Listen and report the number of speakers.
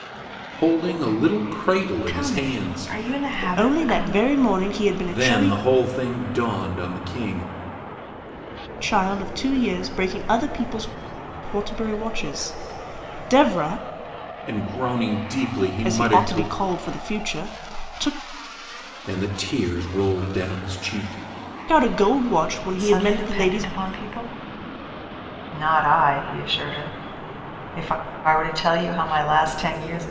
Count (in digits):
3